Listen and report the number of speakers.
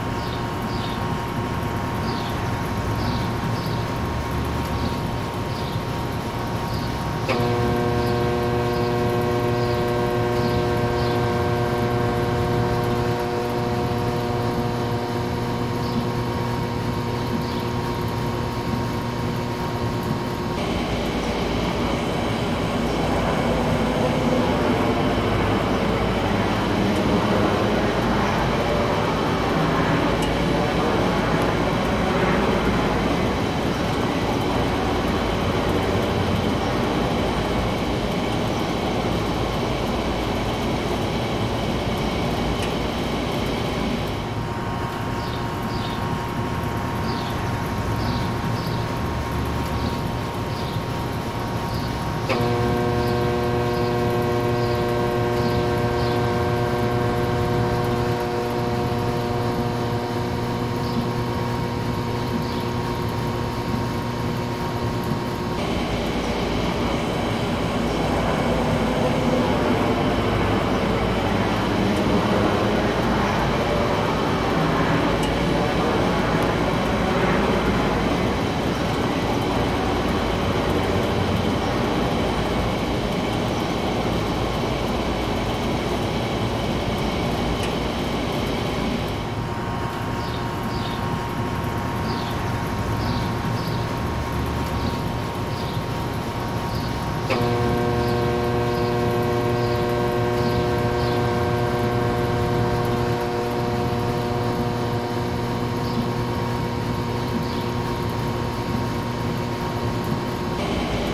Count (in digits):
0